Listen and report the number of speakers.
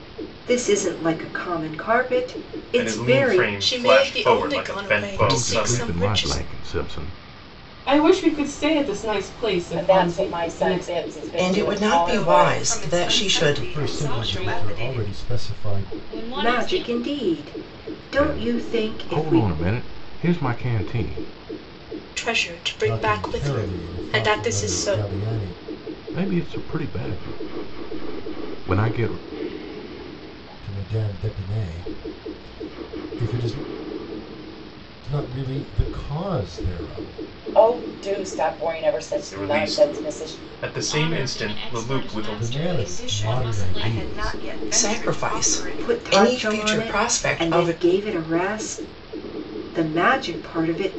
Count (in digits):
10